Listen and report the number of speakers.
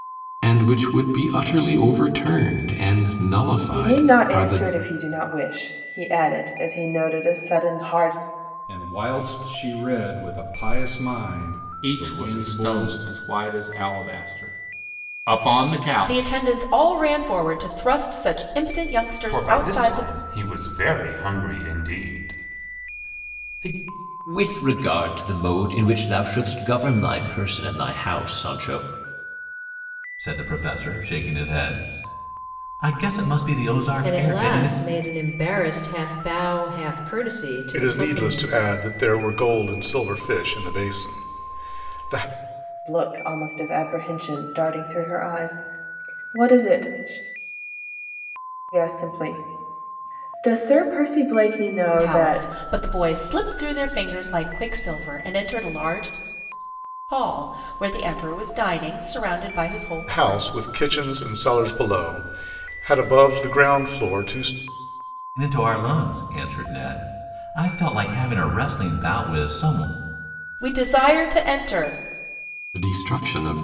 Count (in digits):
10